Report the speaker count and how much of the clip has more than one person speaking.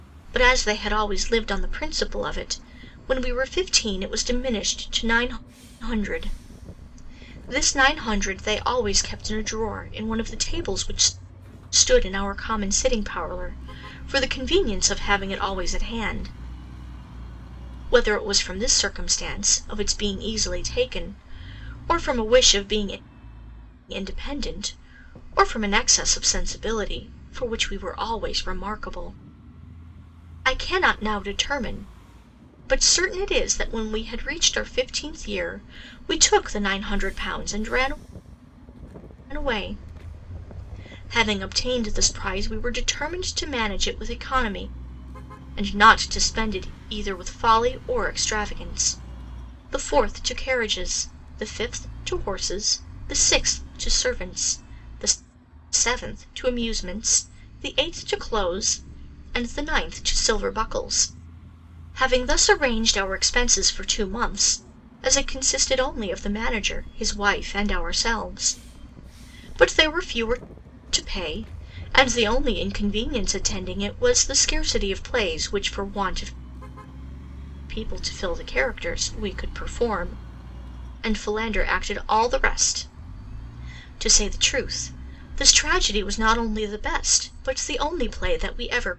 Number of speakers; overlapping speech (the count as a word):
one, no overlap